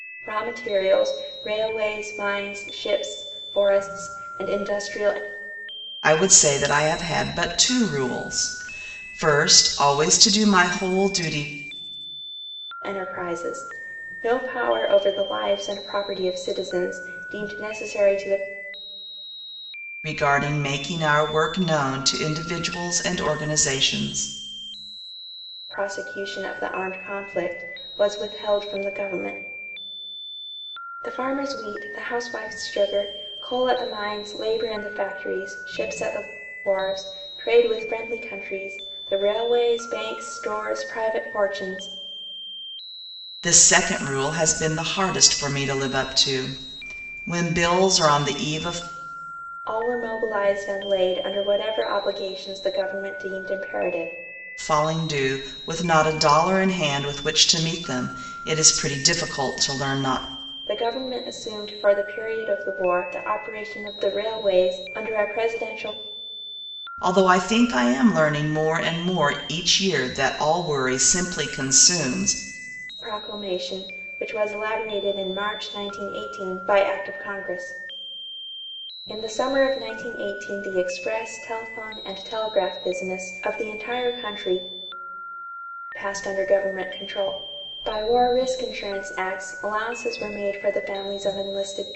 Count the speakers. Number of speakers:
2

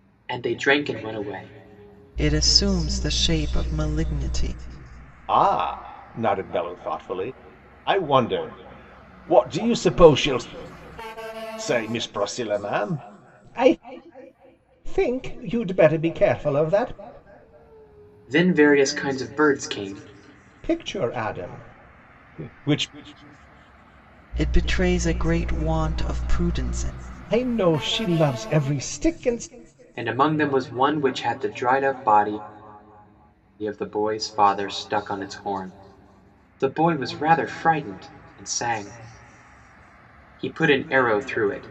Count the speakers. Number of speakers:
3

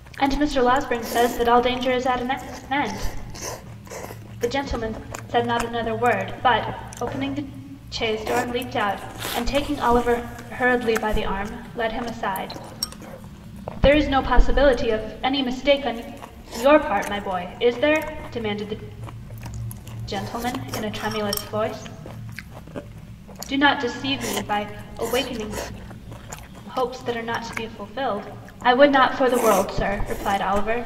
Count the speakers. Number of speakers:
1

